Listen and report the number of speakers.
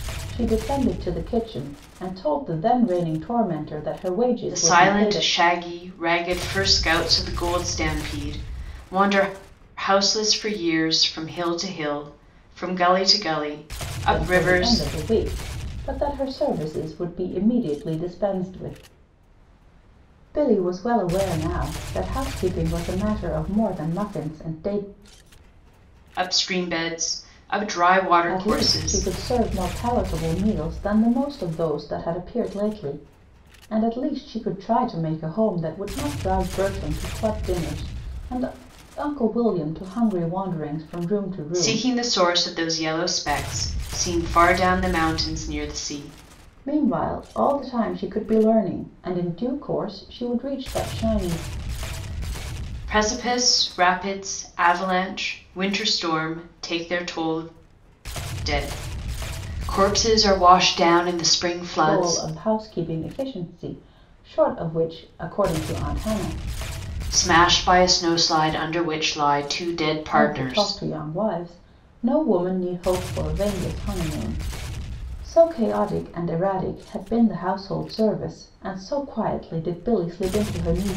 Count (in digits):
2